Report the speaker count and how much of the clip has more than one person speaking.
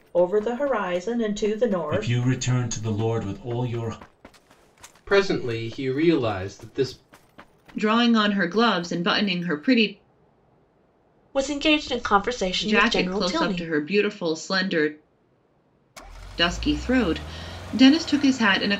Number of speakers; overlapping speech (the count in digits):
5, about 8%